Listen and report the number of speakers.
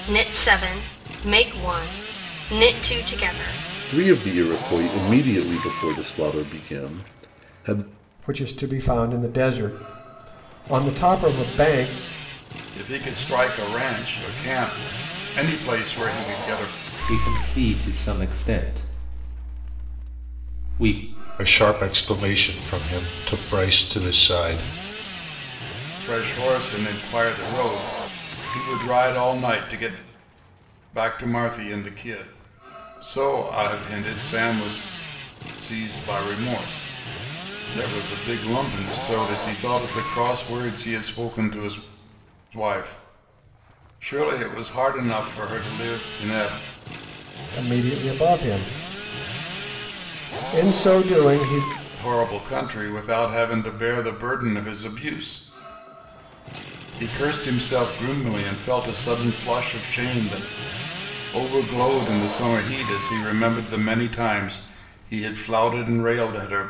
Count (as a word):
six